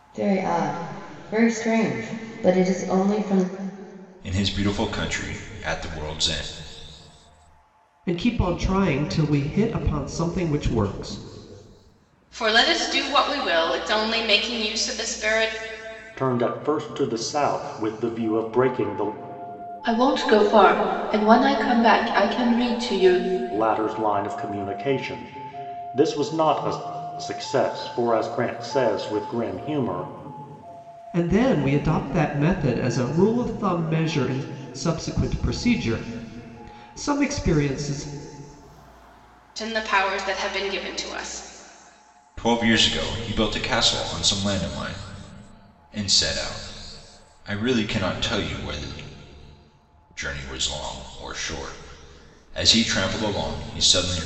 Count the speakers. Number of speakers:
six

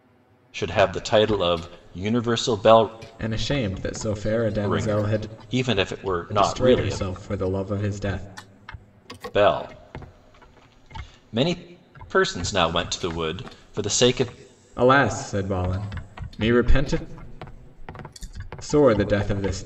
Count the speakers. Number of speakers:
two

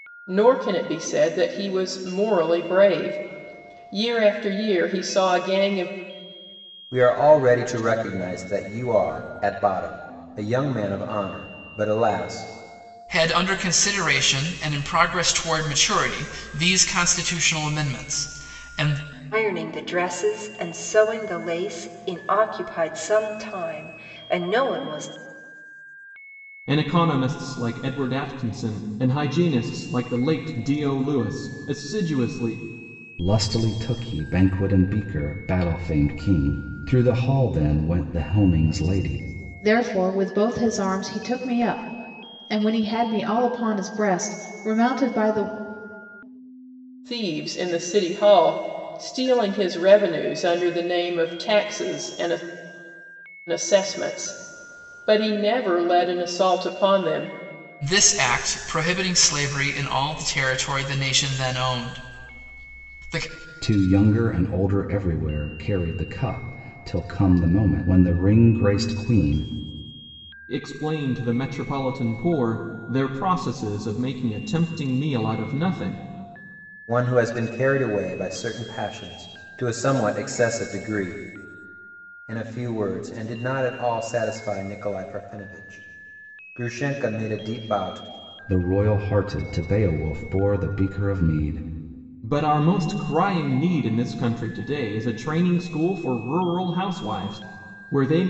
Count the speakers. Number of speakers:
seven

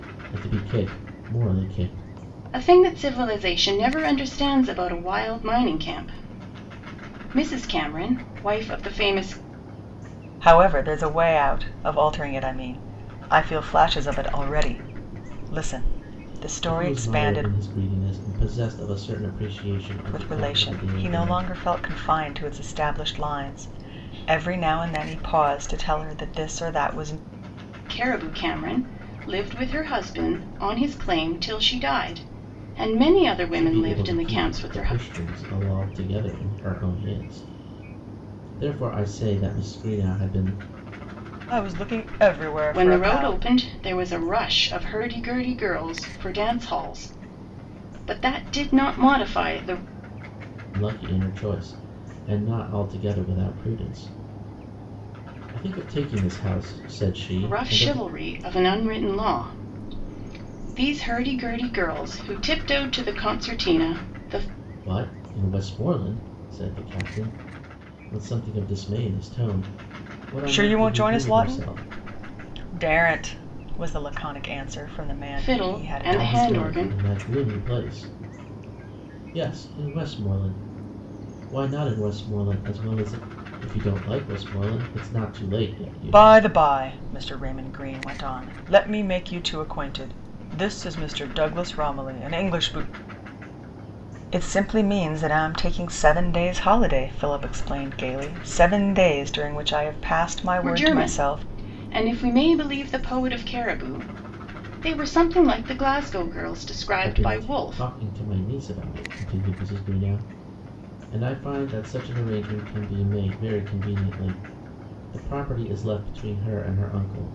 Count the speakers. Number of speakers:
three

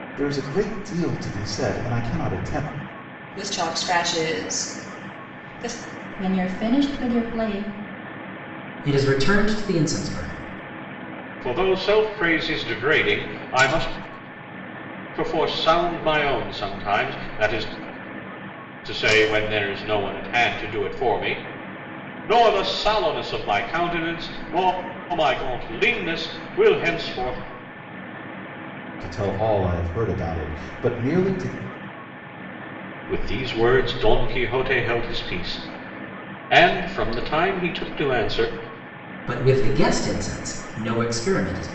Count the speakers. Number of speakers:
five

